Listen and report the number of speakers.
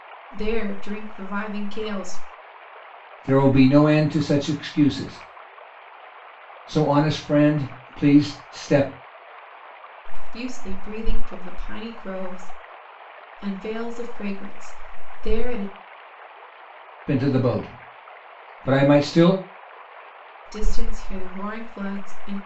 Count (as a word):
two